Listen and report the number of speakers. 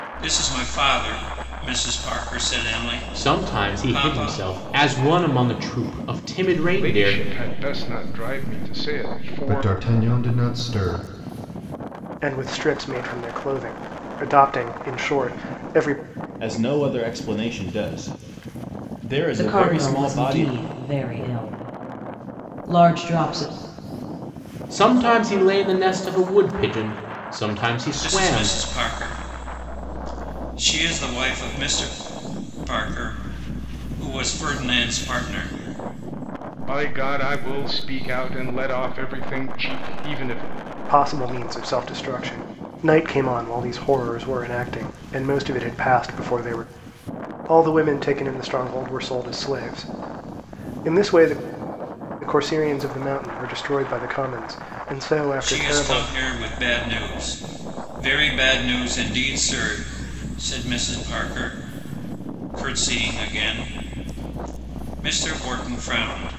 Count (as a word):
seven